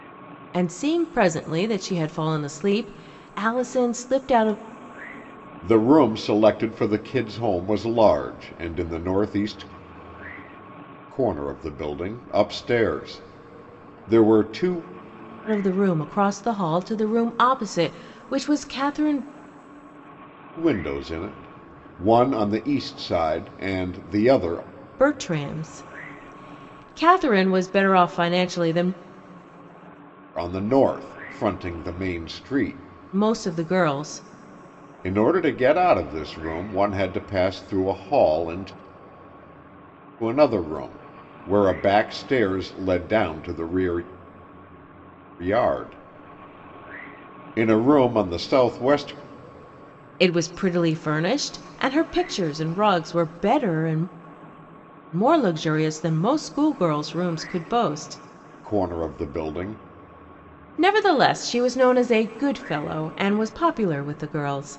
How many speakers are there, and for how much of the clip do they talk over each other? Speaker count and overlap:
two, no overlap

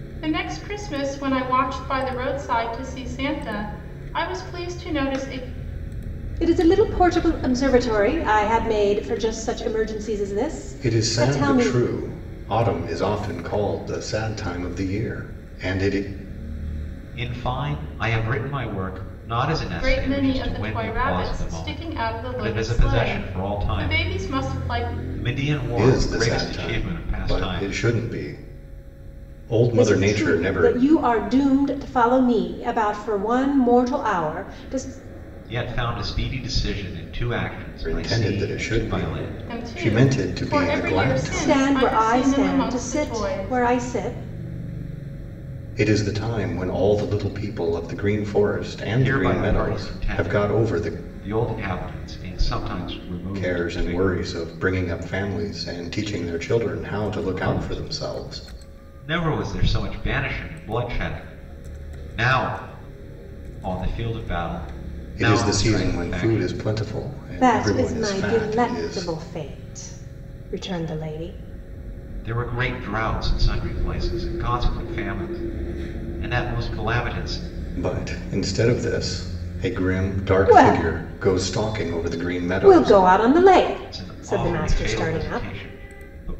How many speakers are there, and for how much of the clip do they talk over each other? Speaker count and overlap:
four, about 31%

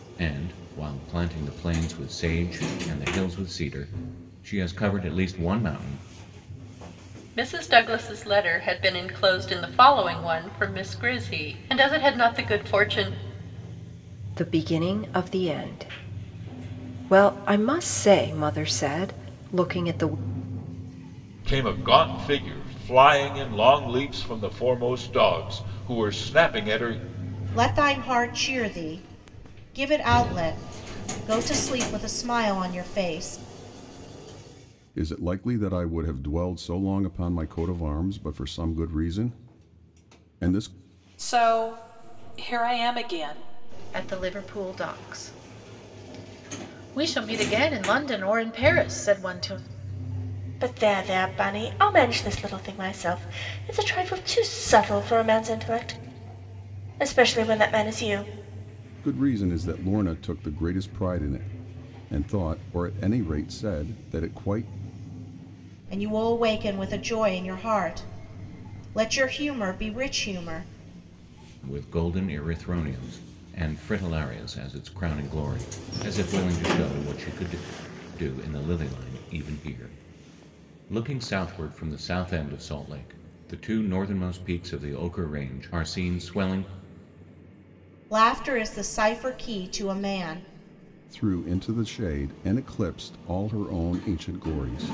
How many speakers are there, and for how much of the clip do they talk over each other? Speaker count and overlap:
nine, no overlap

